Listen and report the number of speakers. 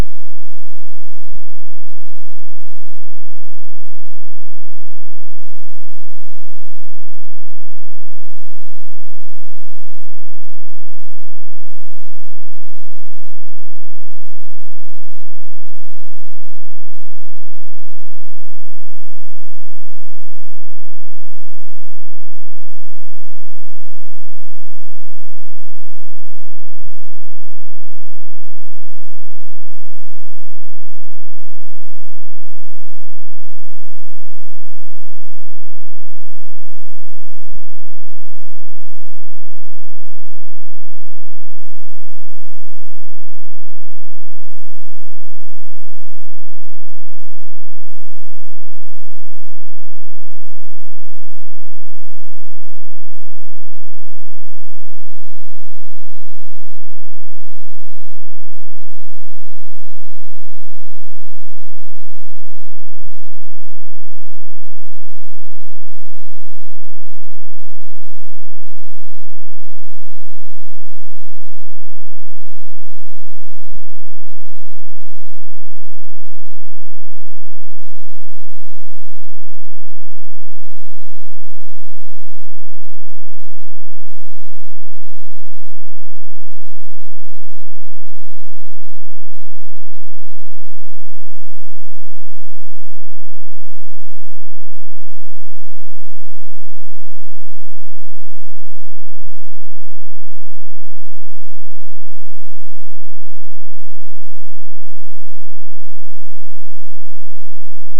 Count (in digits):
0